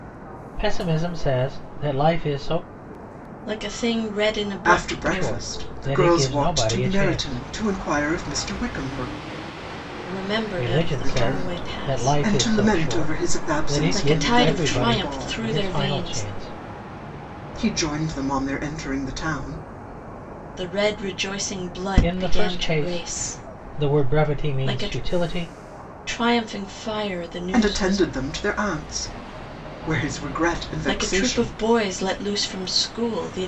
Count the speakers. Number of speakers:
3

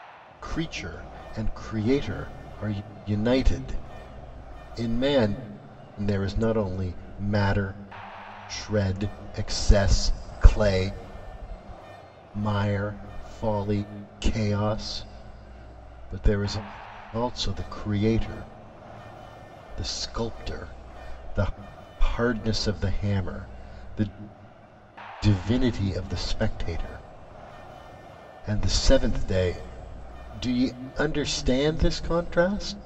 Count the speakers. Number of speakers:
1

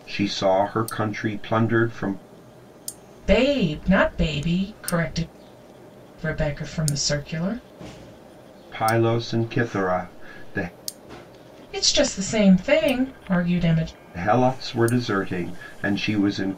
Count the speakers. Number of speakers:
2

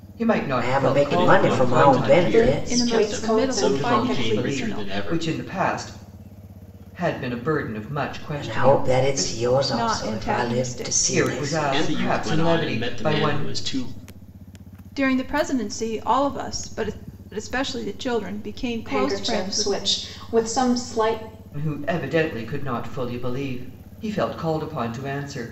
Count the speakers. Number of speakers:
5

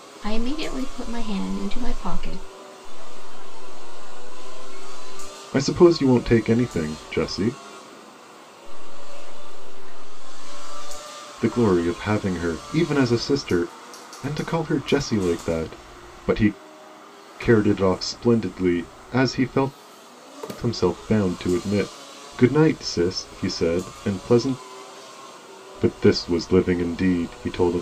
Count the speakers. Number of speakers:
3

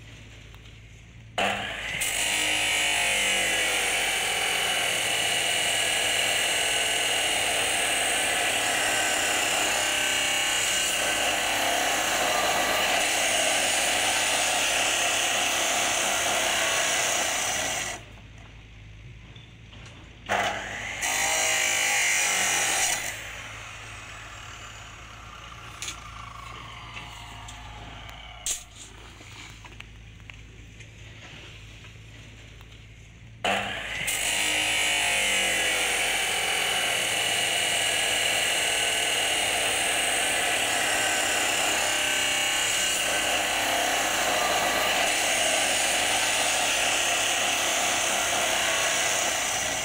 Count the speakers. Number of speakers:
0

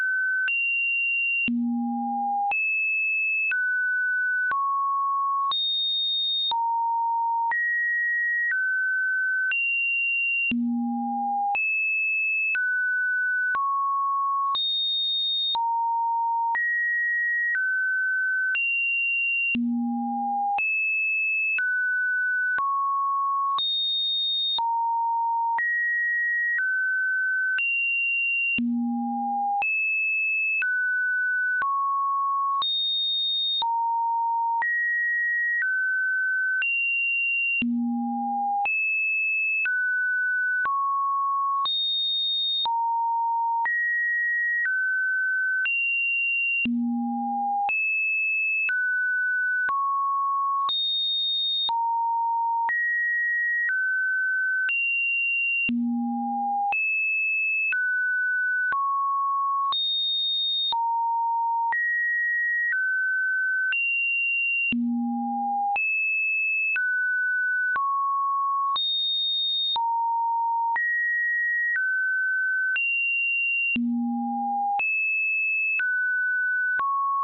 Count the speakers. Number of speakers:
0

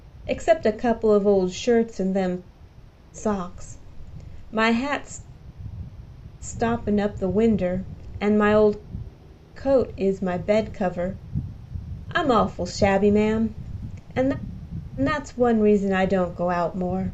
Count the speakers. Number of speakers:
1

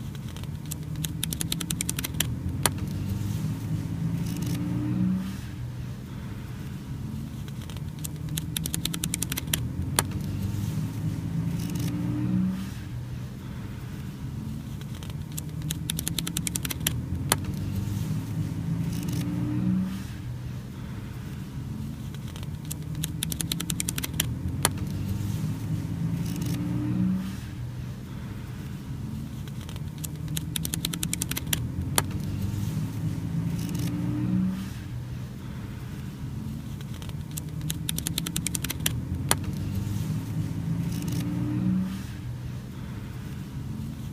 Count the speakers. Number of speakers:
0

